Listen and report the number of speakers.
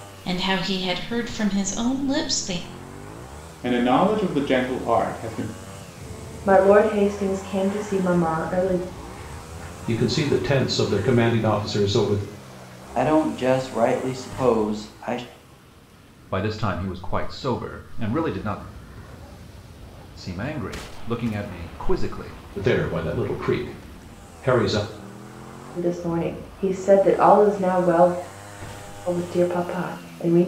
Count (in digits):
6